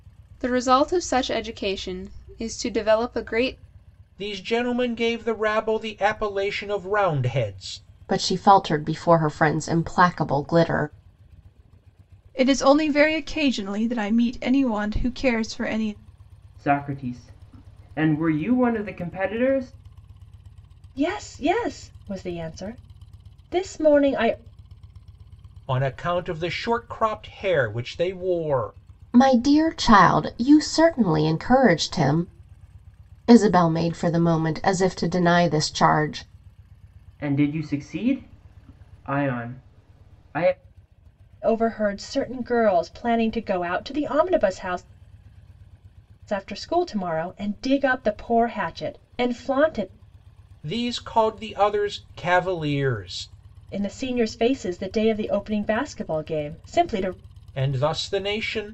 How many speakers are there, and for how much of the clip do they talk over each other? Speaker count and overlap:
6, no overlap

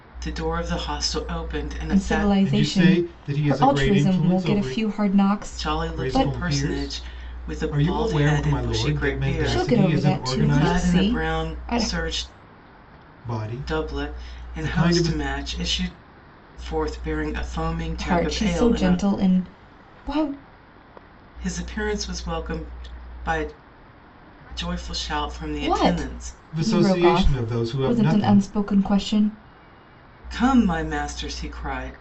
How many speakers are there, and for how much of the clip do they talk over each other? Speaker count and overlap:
3, about 45%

